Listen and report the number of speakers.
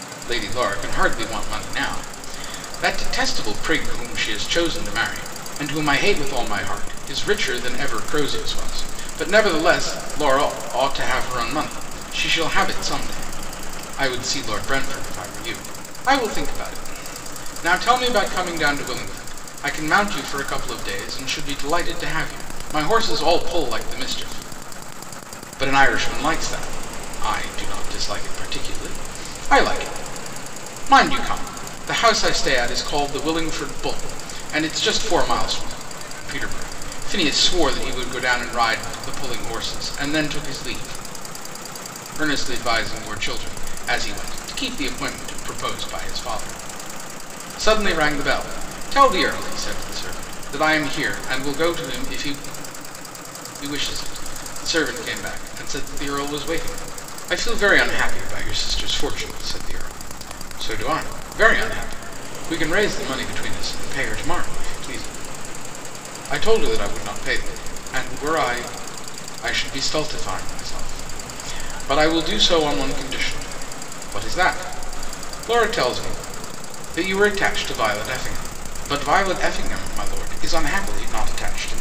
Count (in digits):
1